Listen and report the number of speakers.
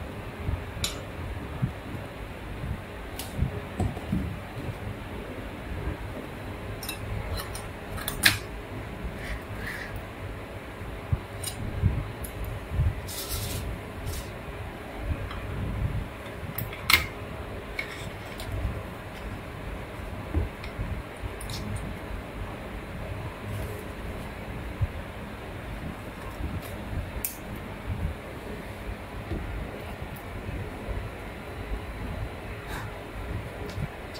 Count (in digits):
0